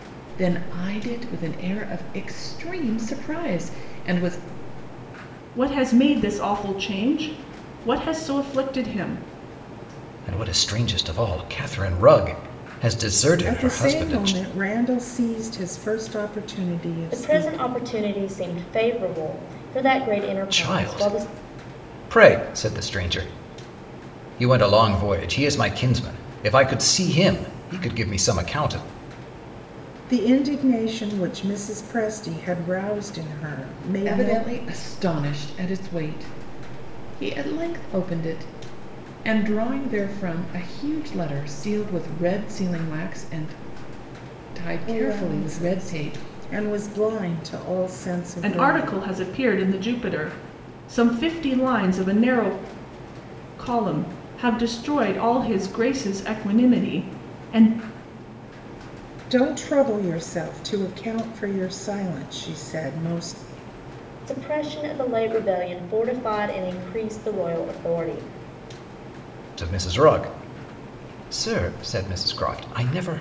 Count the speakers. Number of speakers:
5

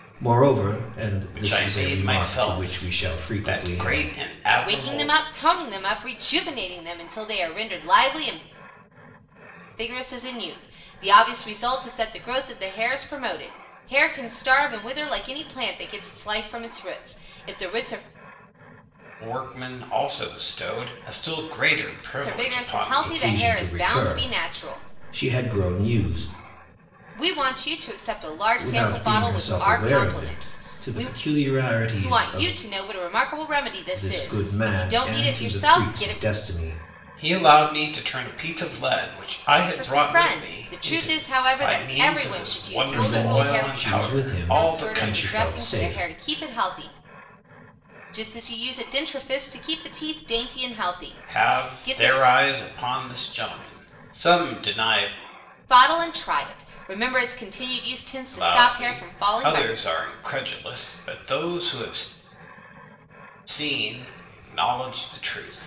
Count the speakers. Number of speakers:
3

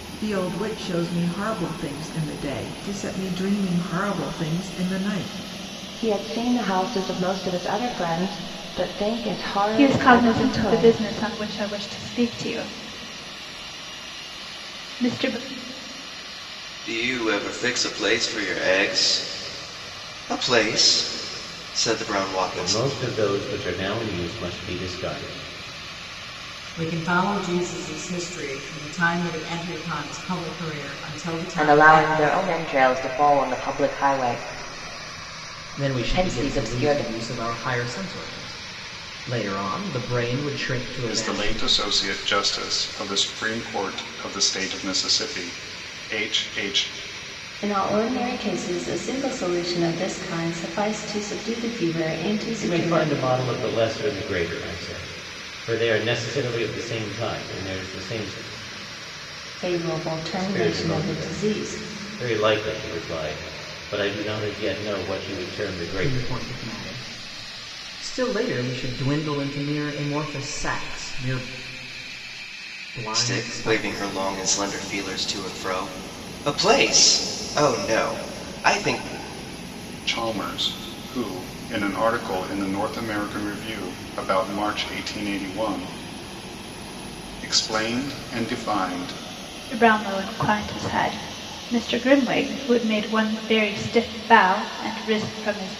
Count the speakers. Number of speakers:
10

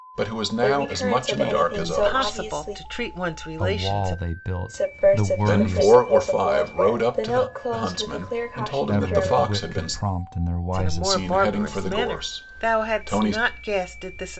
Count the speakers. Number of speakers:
4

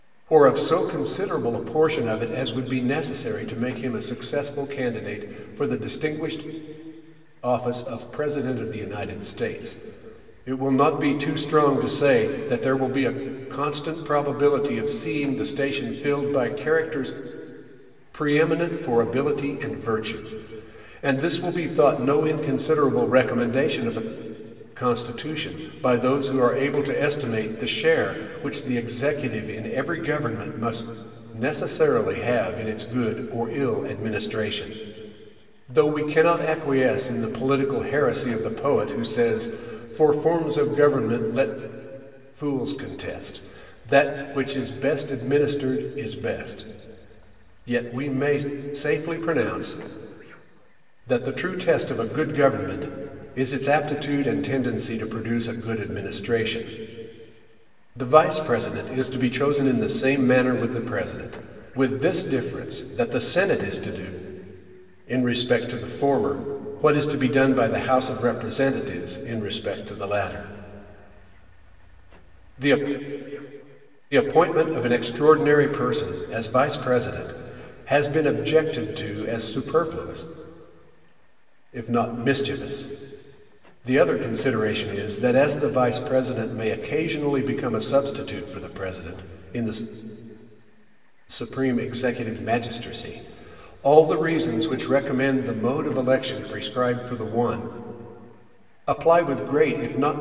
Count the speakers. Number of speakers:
1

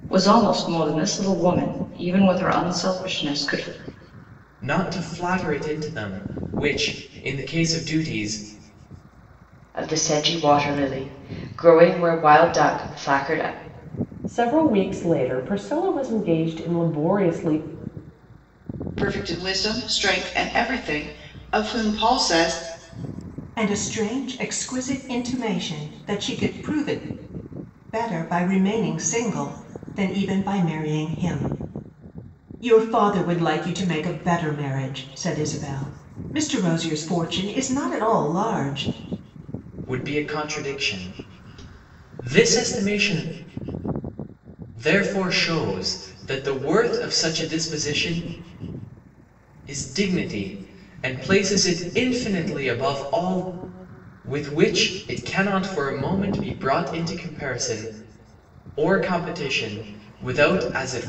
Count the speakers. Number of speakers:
6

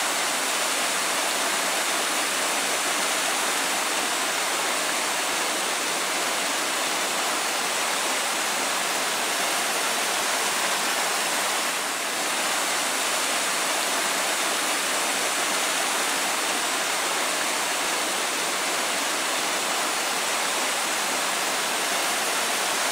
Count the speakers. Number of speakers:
0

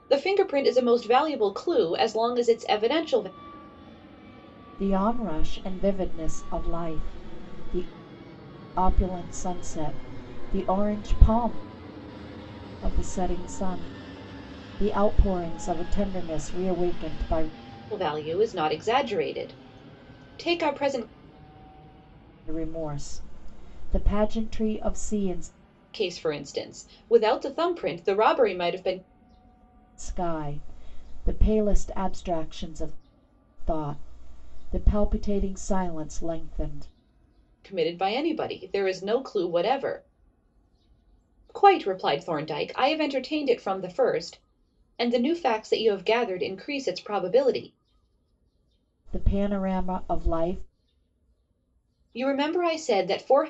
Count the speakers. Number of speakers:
2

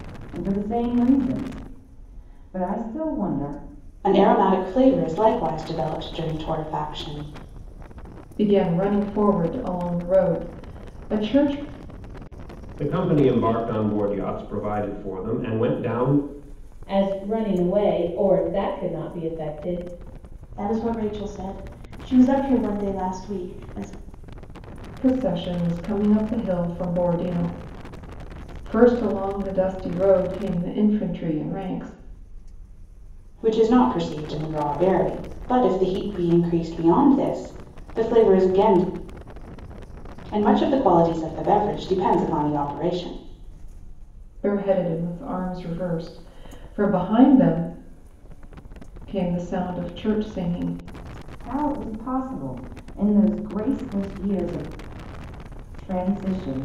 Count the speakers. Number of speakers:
6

